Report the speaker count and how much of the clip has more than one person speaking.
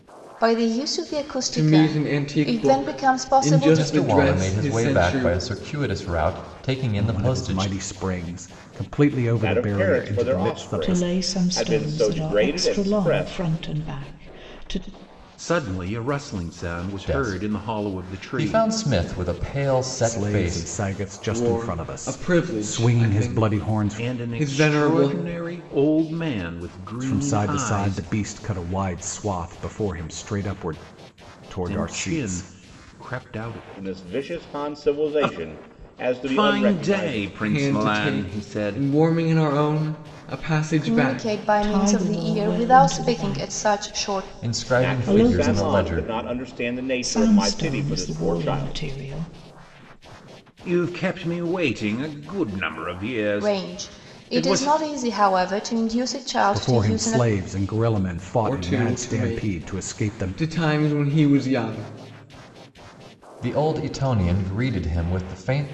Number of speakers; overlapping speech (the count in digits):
7, about 49%